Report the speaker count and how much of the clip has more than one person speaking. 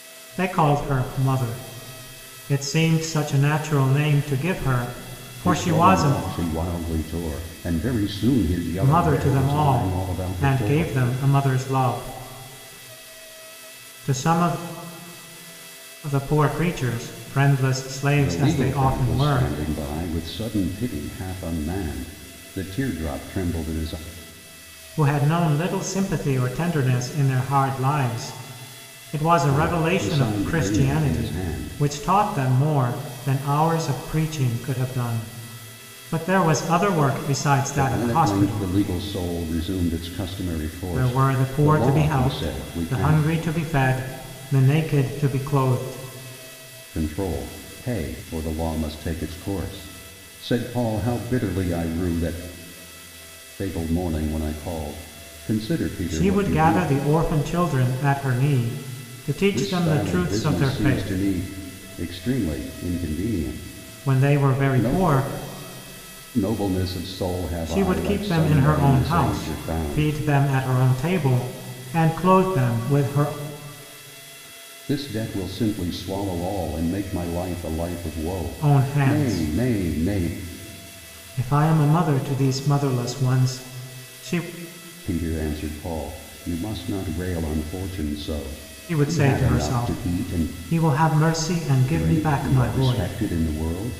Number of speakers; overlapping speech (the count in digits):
2, about 22%